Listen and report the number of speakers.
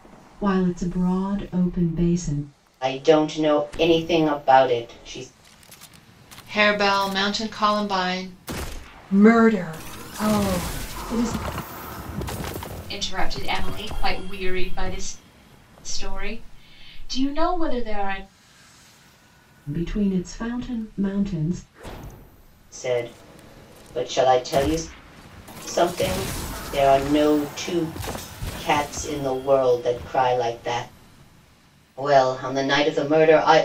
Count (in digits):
5